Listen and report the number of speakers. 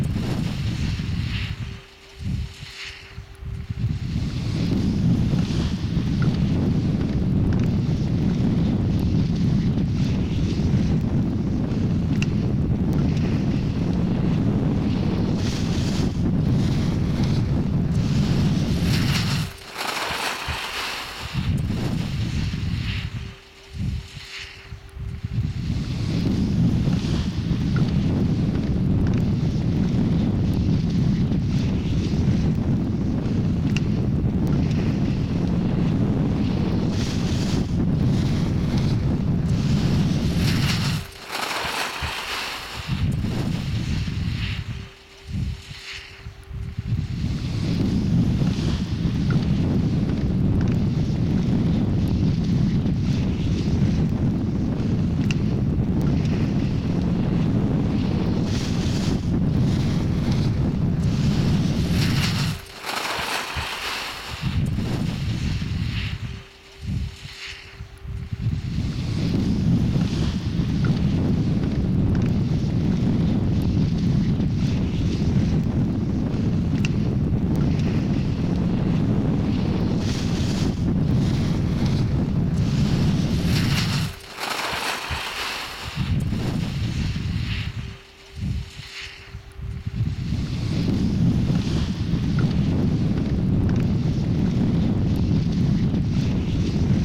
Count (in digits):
0